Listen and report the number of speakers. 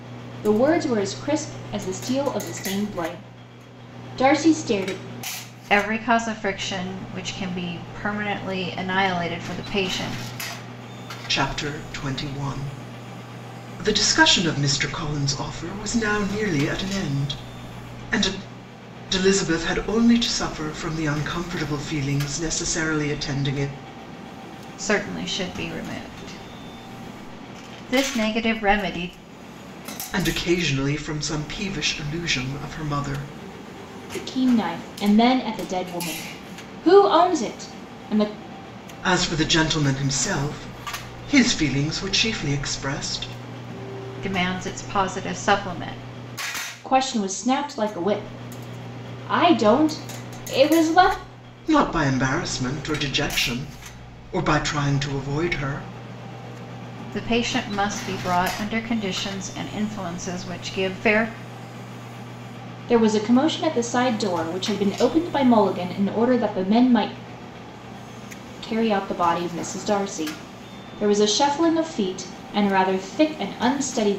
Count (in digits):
3